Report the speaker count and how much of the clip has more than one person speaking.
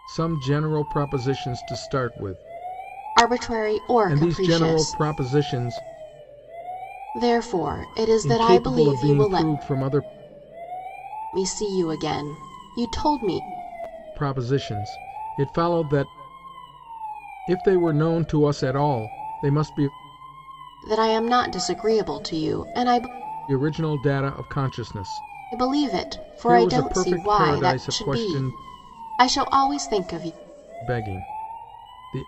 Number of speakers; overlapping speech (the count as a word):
two, about 14%